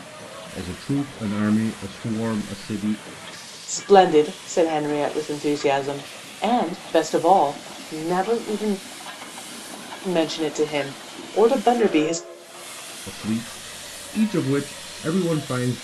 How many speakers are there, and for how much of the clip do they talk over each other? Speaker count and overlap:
two, no overlap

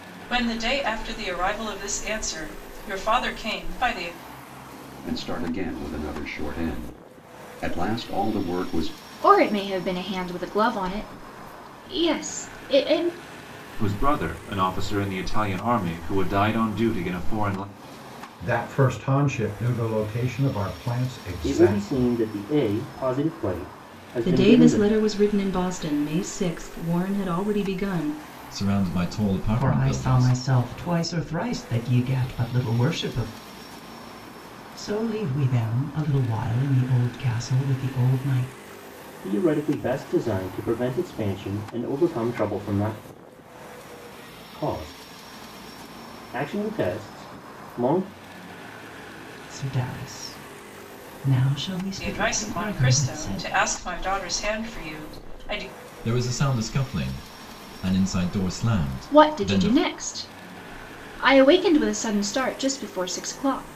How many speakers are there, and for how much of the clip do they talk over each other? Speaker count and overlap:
nine, about 7%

